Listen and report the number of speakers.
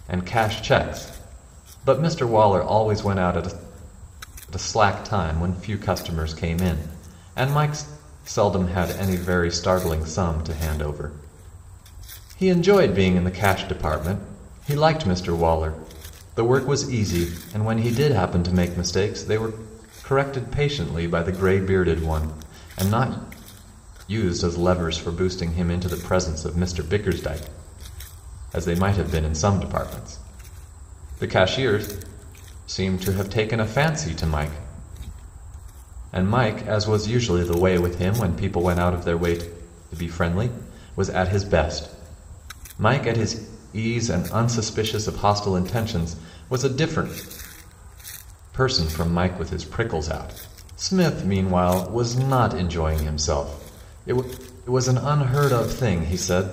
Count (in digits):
1